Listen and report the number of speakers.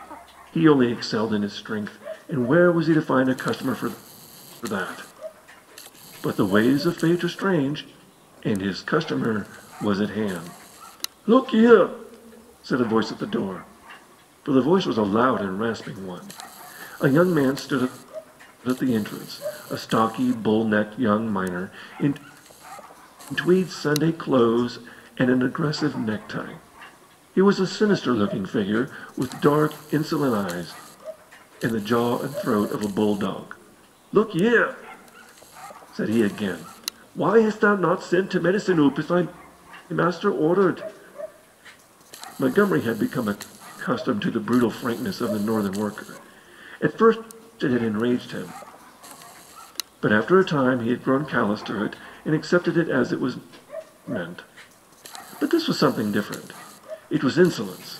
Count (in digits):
1